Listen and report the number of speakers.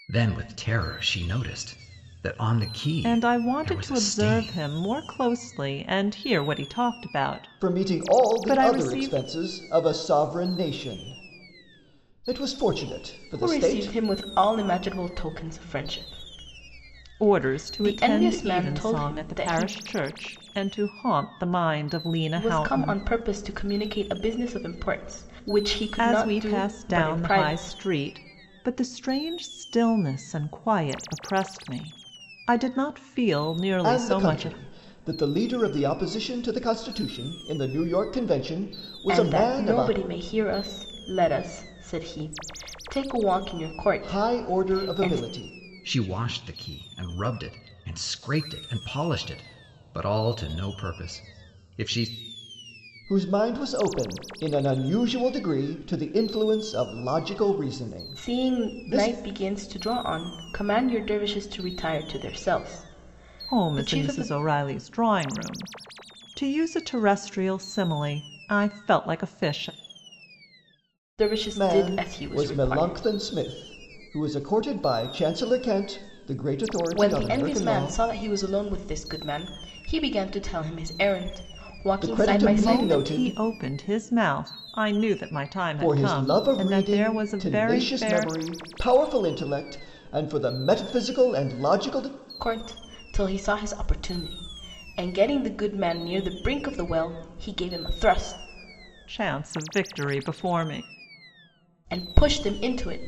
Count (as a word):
four